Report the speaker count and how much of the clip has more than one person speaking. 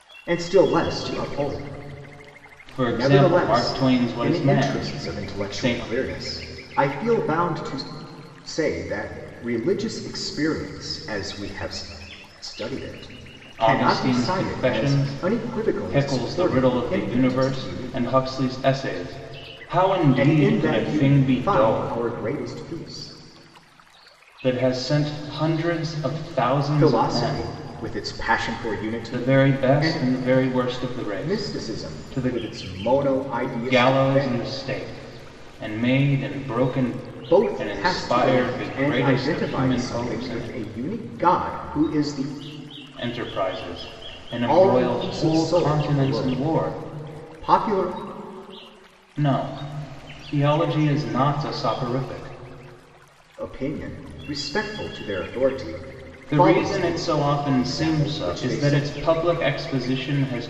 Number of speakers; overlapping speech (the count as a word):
two, about 34%